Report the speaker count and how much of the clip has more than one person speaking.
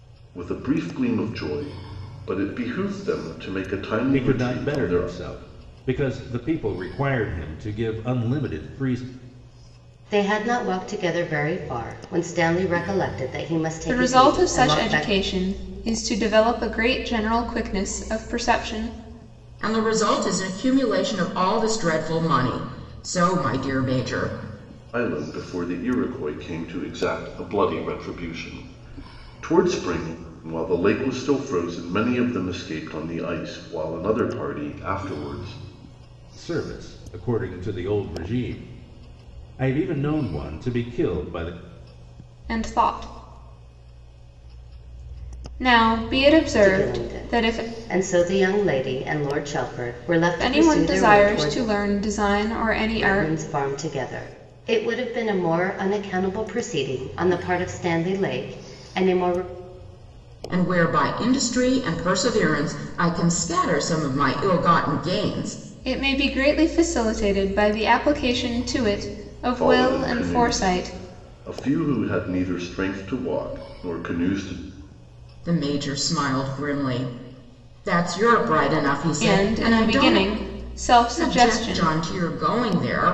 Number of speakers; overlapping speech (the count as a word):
five, about 10%